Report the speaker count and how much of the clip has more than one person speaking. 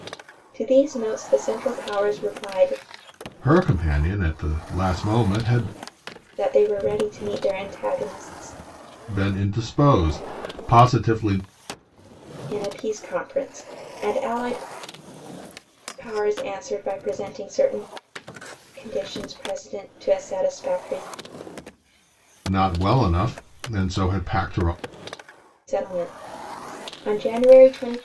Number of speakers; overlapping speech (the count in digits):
2, no overlap